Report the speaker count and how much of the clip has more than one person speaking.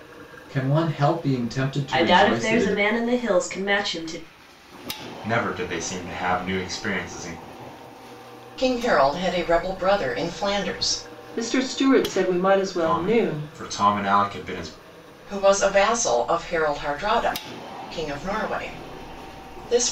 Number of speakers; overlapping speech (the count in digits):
5, about 8%